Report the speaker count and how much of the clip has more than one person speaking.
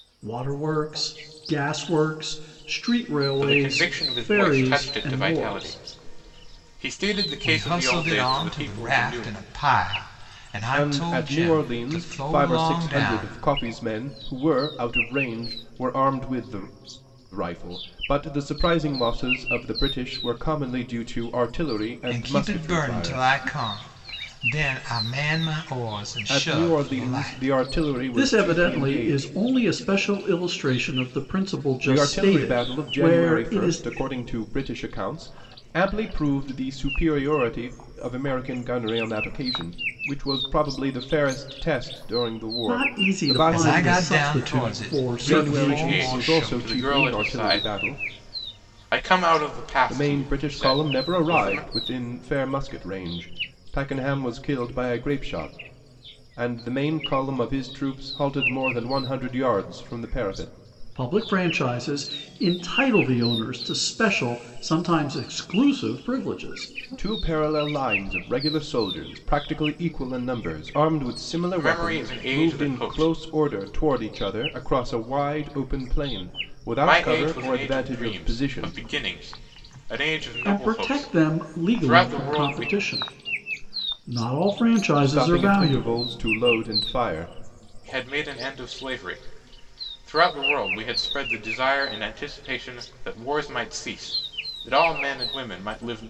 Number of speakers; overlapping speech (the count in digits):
4, about 28%